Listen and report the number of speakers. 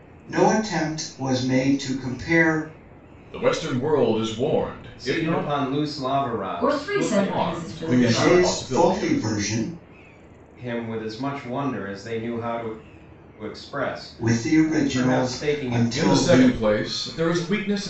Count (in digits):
4